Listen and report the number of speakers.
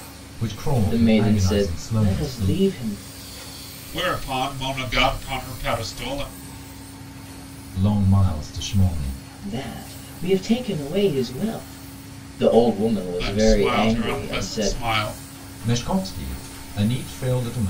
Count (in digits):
3